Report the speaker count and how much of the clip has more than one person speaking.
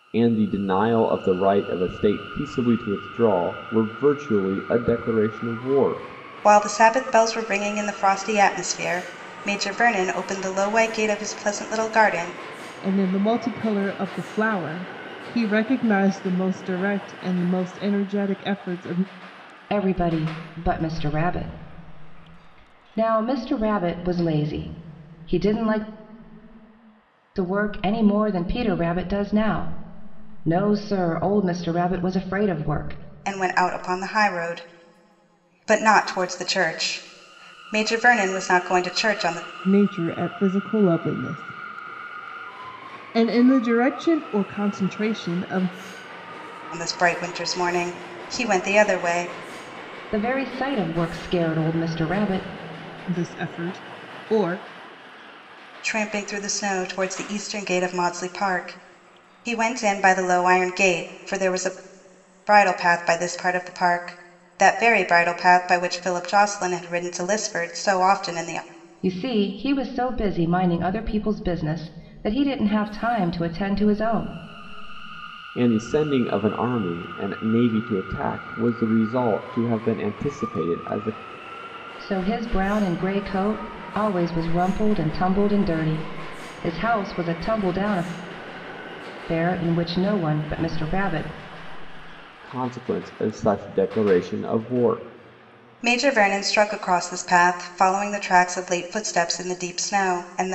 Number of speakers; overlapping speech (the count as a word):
four, no overlap